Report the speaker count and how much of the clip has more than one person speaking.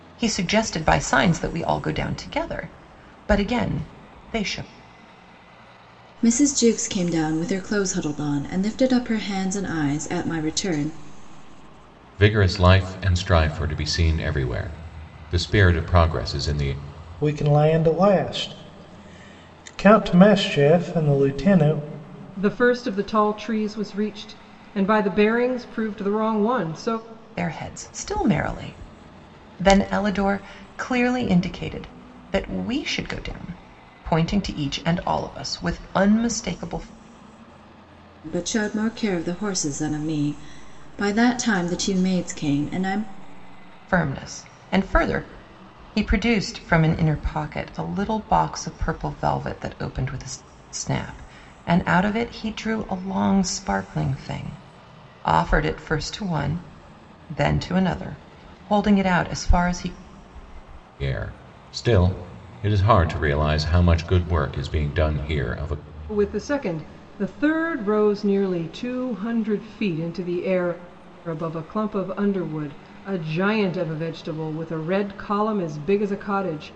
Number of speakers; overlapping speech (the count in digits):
5, no overlap